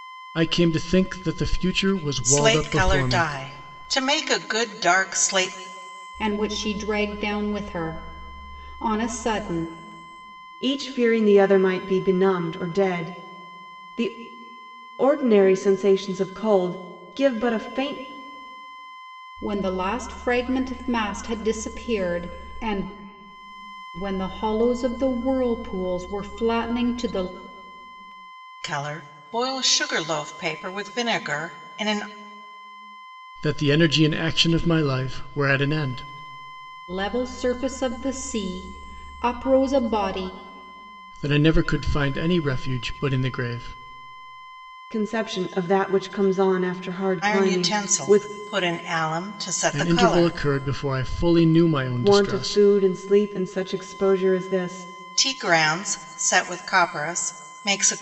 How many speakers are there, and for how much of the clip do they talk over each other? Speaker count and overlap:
4, about 6%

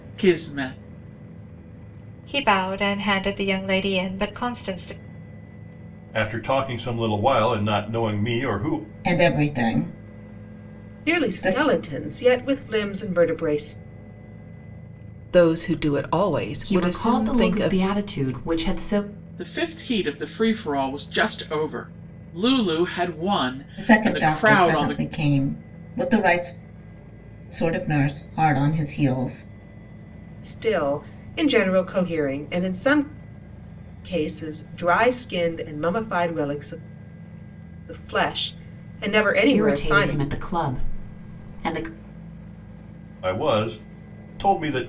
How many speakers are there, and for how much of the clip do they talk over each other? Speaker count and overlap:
7, about 9%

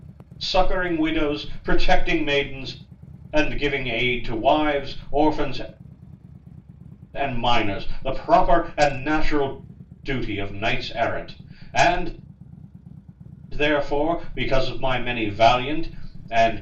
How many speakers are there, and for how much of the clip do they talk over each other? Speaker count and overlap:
1, no overlap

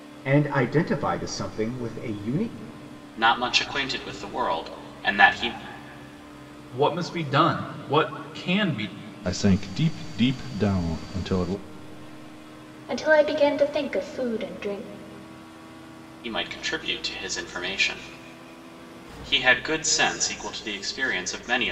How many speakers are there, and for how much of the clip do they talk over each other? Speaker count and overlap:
5, no overlap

